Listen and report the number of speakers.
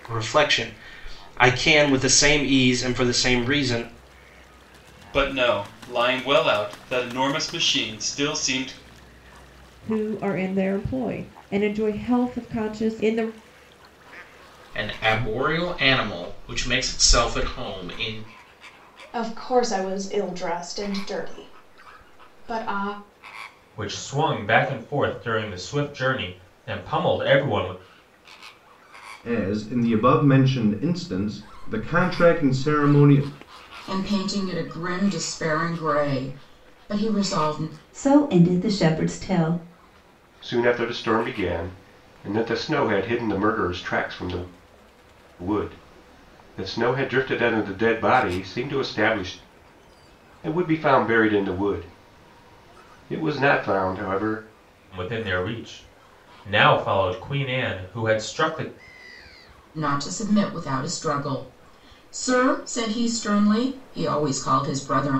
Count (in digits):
10